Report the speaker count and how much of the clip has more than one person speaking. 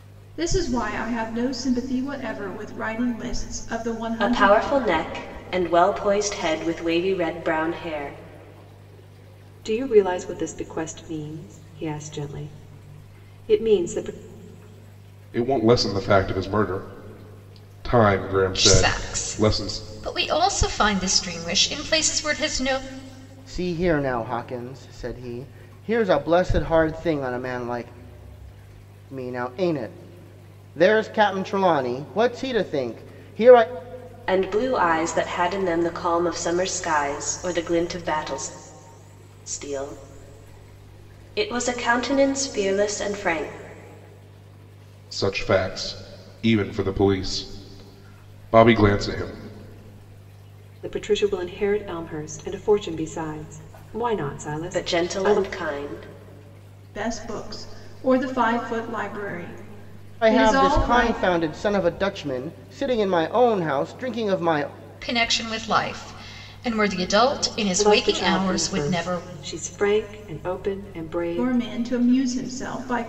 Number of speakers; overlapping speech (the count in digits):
6, about 7%